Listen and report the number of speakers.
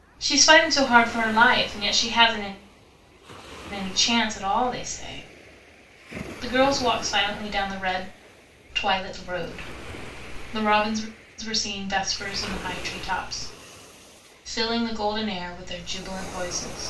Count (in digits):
1